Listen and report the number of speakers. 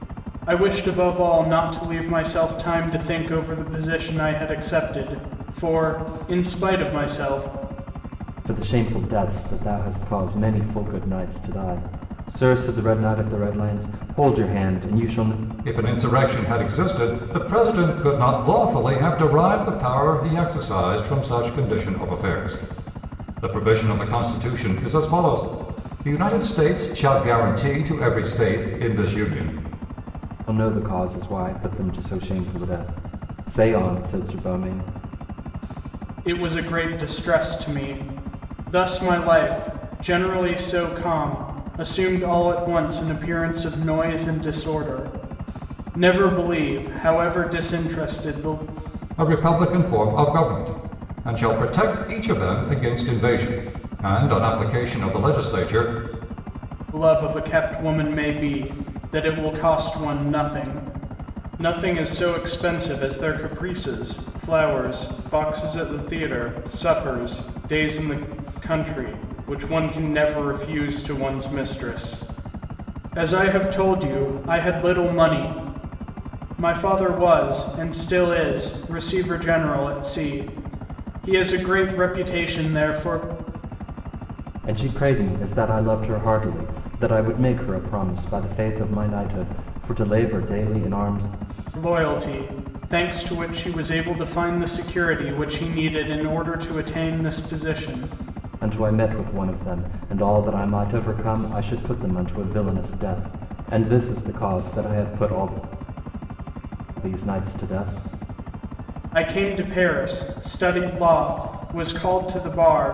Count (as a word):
three